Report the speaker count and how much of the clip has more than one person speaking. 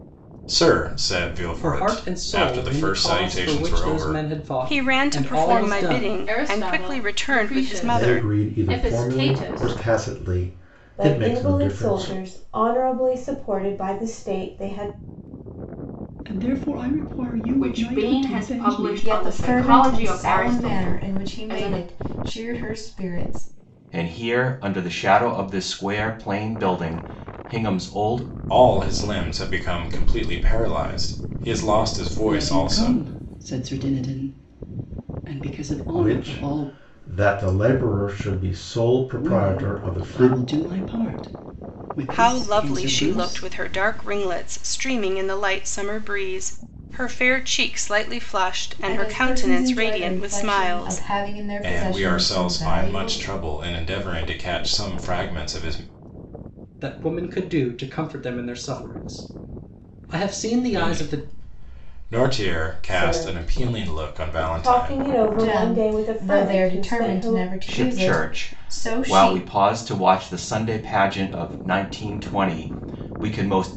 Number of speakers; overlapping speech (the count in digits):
10, about 38%